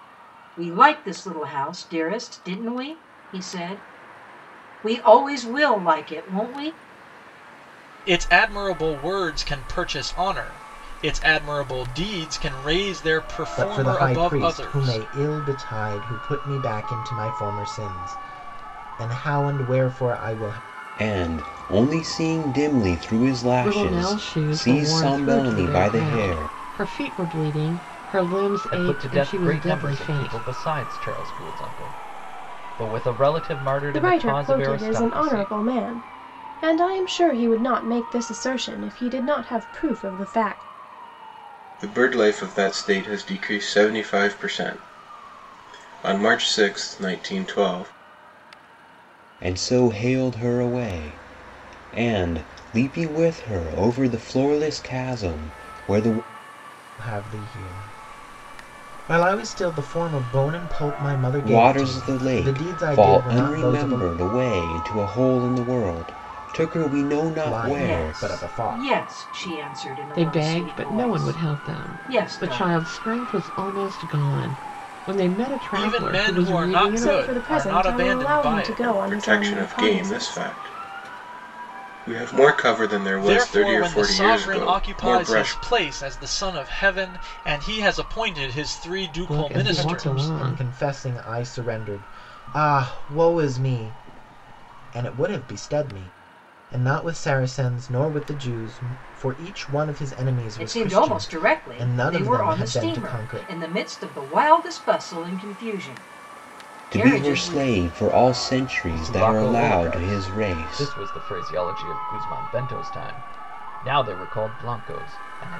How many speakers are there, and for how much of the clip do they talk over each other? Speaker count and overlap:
8, about 26%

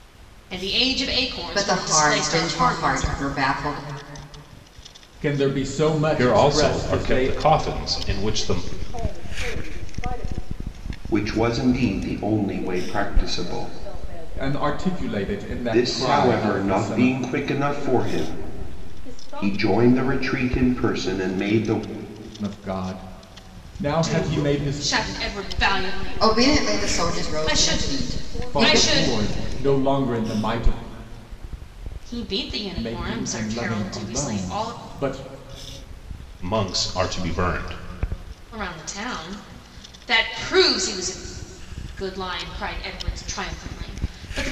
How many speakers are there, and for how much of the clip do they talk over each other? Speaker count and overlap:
6, about 37%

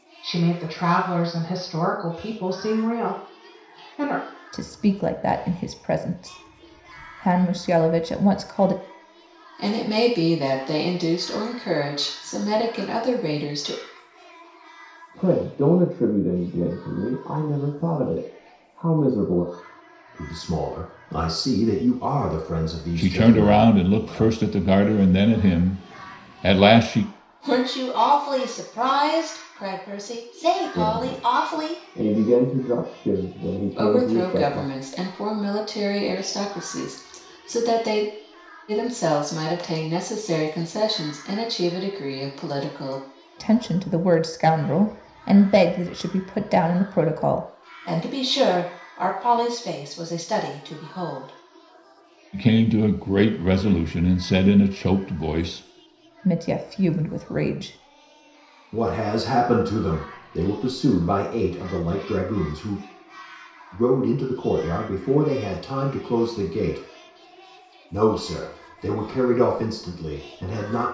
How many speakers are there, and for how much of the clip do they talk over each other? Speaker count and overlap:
7, about 5%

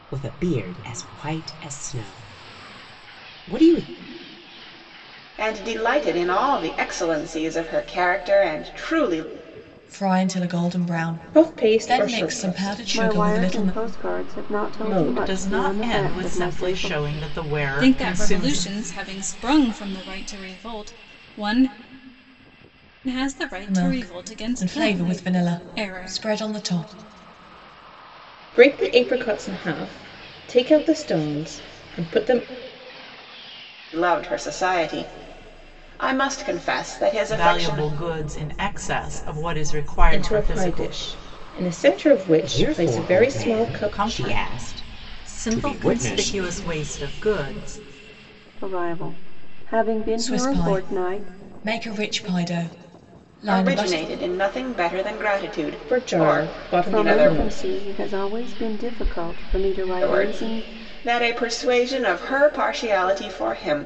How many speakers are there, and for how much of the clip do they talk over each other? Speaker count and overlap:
7, about 29%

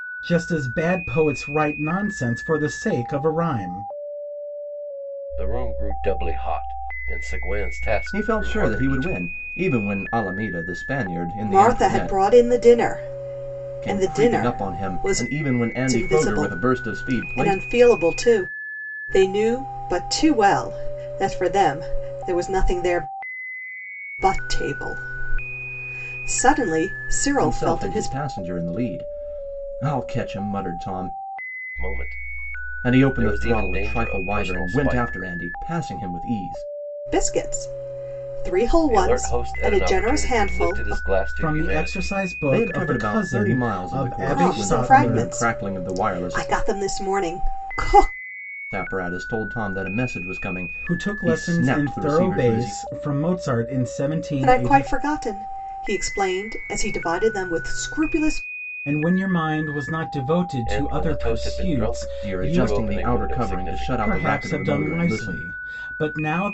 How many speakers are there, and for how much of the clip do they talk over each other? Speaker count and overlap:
4, about 34%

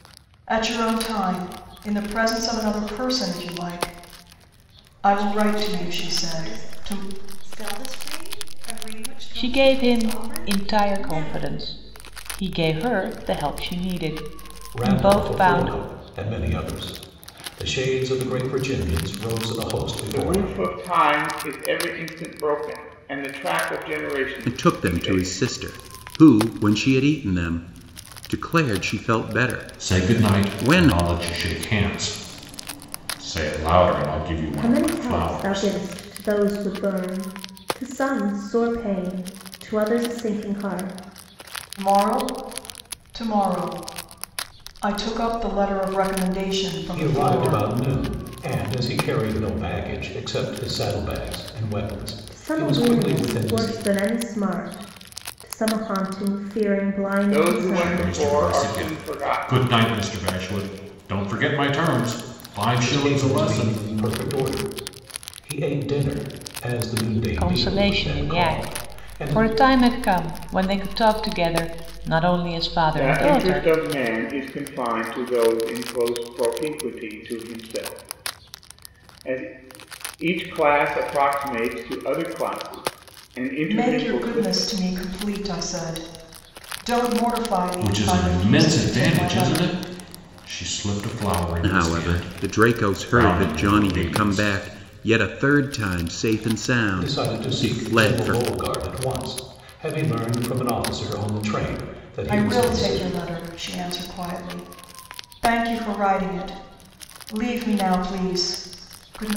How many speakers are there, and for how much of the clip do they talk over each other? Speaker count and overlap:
8, about 24%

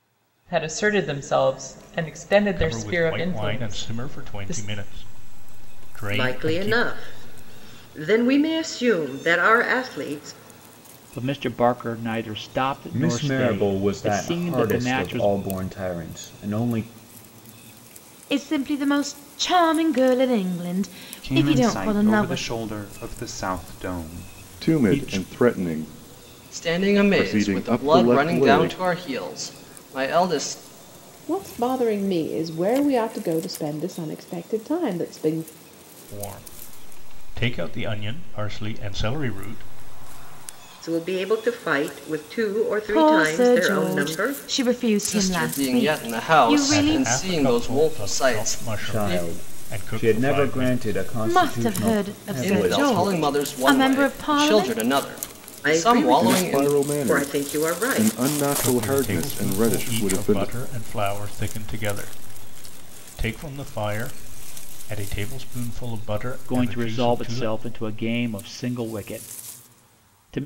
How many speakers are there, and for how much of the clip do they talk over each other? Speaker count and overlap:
10, about 38%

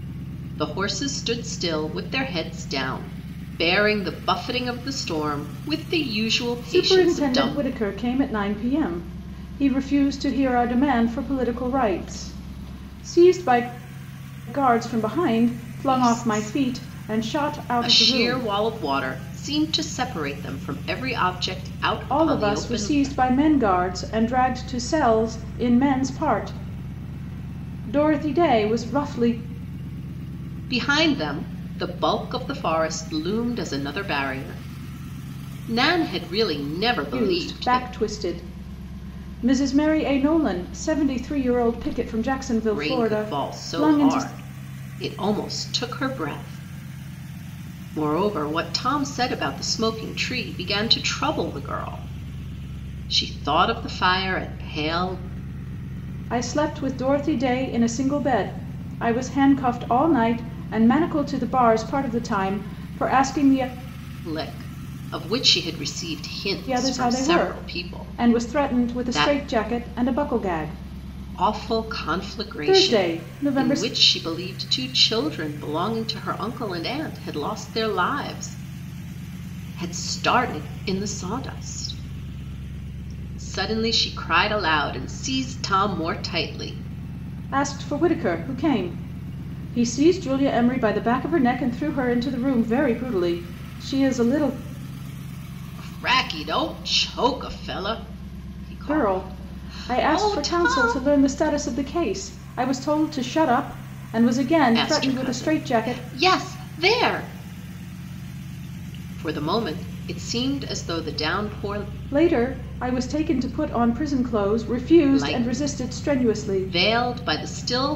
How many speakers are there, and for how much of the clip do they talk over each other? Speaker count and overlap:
2, about 15%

